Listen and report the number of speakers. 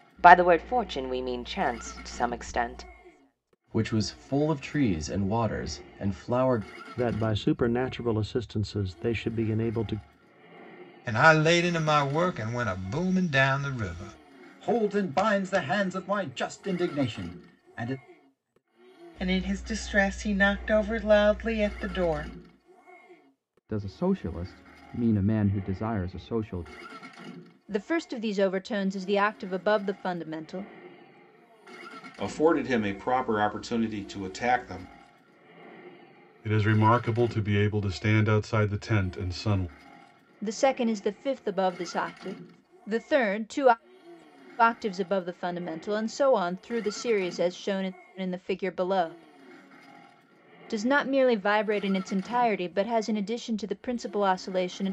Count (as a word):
ten